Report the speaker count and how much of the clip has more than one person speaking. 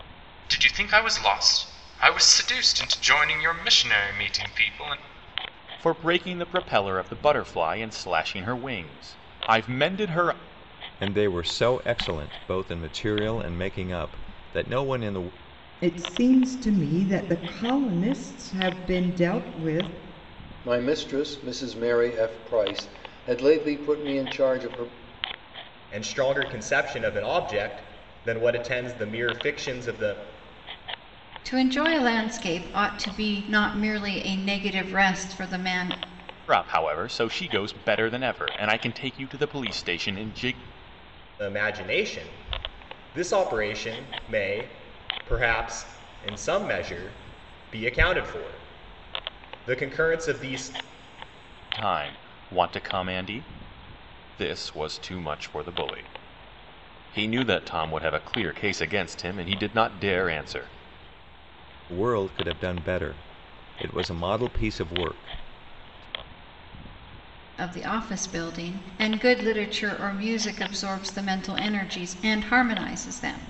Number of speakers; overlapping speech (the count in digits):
7, no overlap